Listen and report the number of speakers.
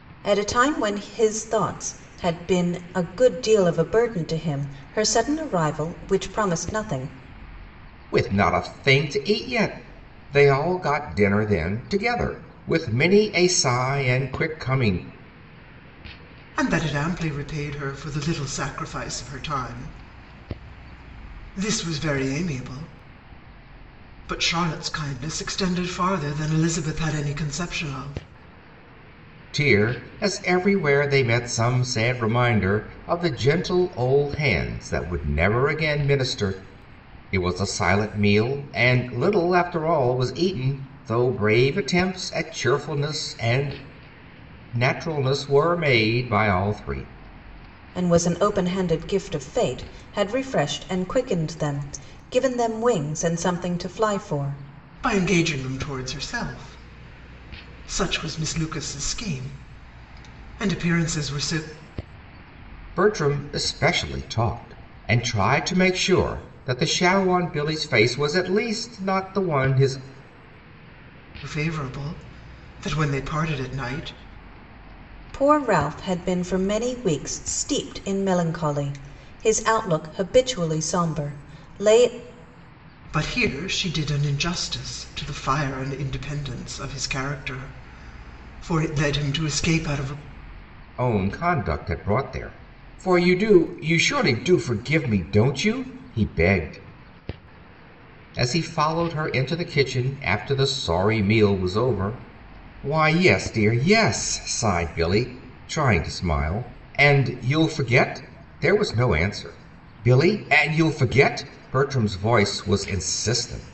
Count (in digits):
3